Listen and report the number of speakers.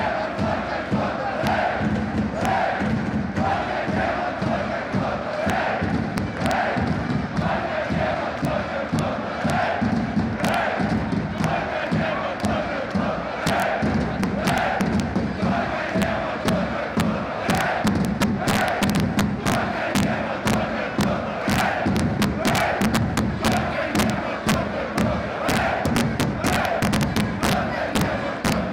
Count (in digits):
0